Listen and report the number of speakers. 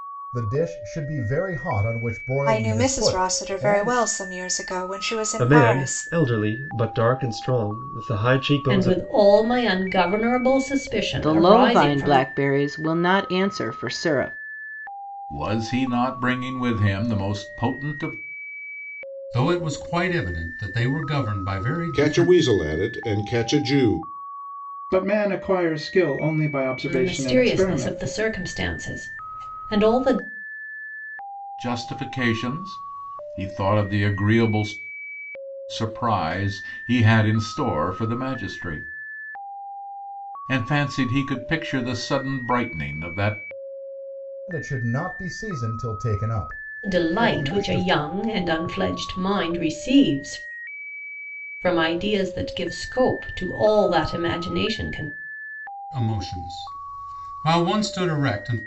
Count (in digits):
9